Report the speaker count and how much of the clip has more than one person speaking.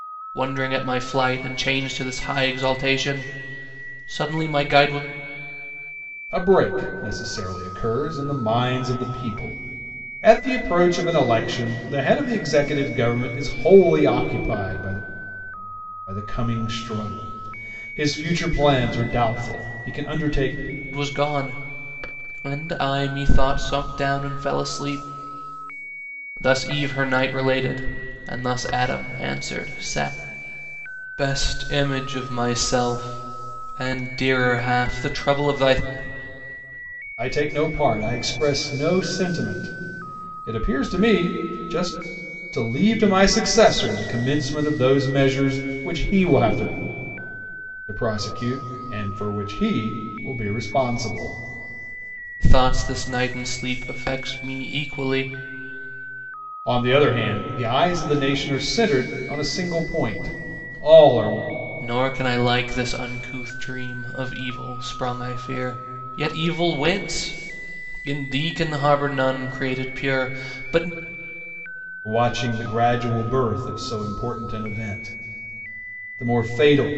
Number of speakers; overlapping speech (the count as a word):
two, no overlap